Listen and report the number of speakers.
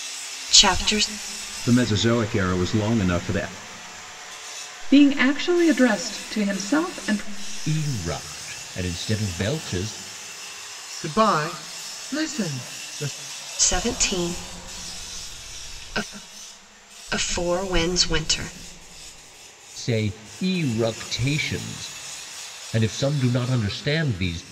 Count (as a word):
five